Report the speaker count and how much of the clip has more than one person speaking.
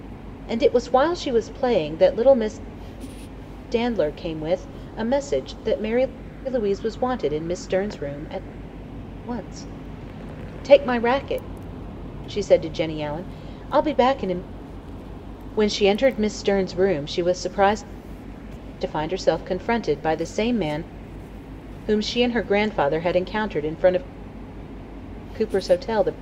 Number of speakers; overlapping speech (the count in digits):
1, no overlap